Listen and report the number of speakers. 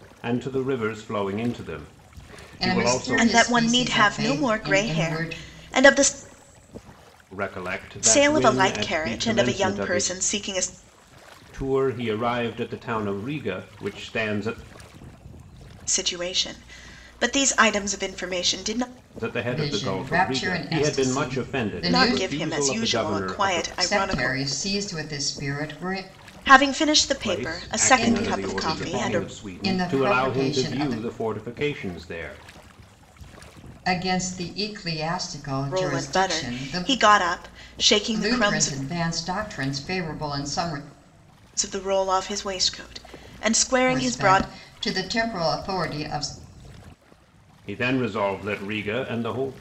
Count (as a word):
three